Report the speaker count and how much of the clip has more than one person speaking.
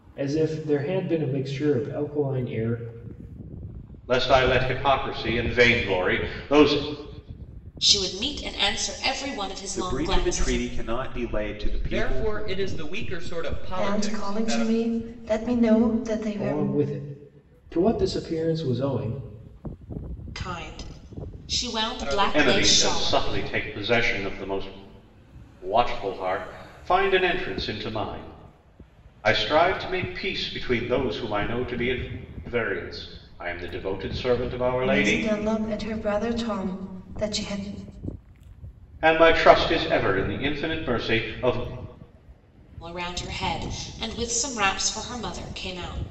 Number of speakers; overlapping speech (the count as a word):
six, about 10%